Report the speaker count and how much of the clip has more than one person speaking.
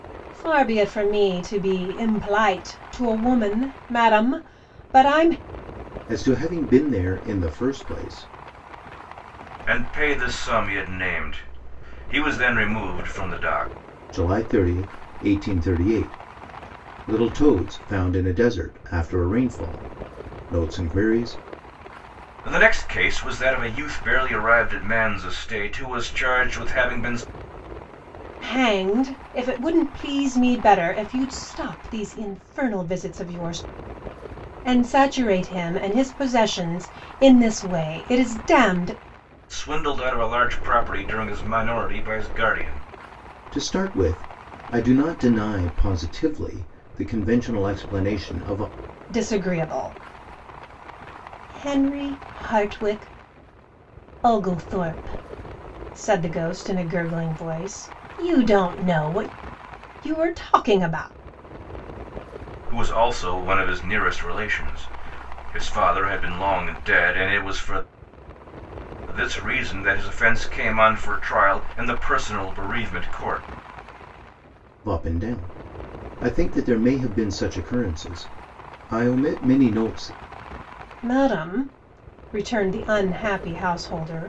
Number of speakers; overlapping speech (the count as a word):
three, no overlap